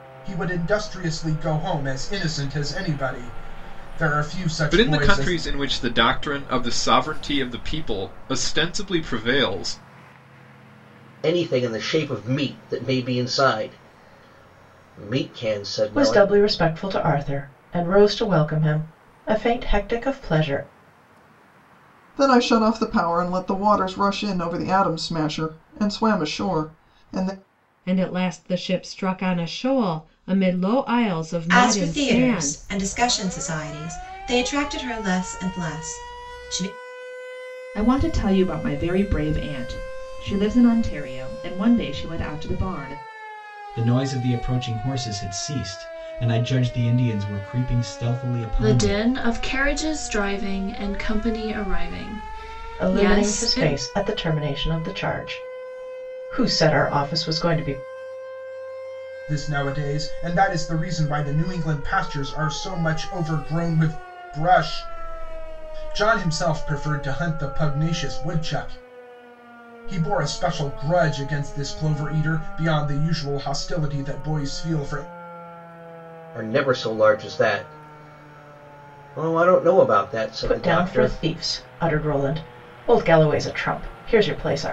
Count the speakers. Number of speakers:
ten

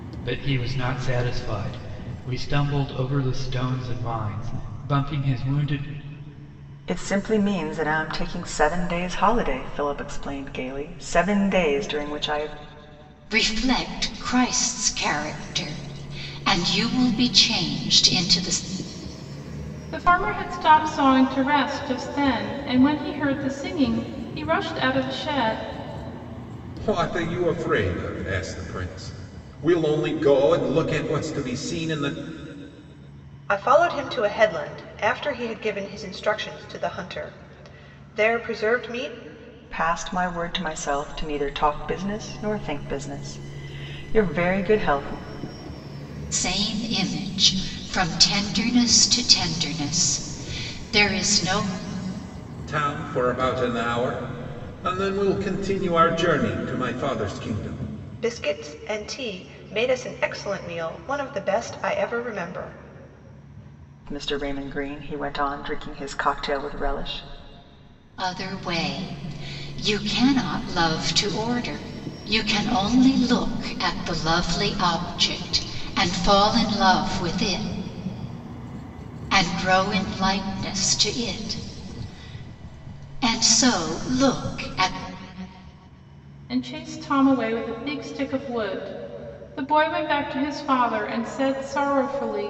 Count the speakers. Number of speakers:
six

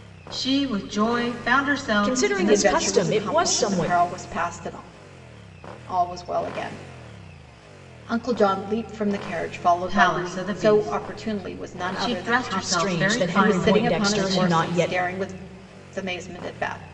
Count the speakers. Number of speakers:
three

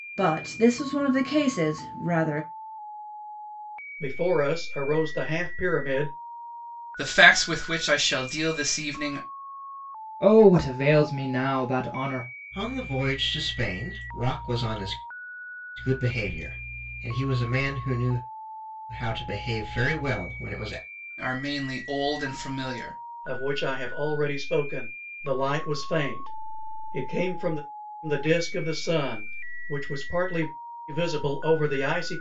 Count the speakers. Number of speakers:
five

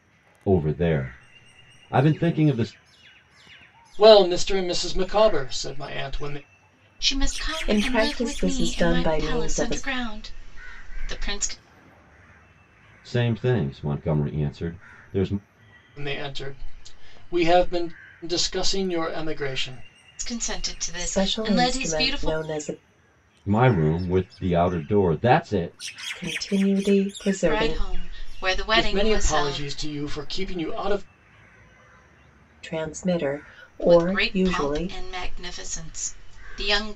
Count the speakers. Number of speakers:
four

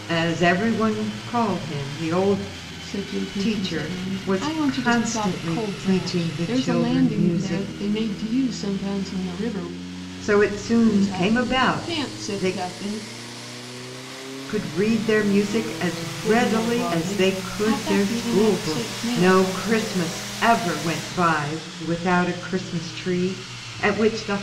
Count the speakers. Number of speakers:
two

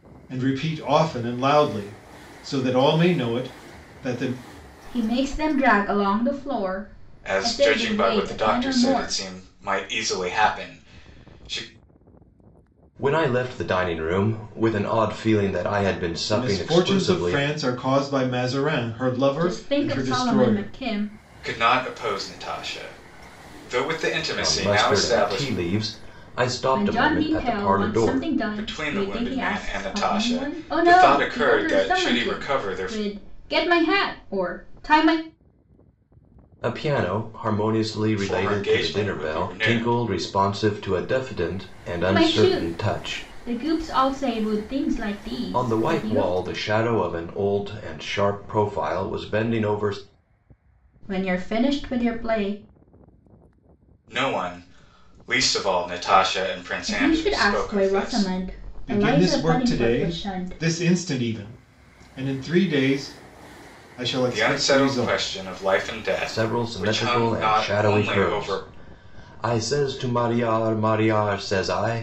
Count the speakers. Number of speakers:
four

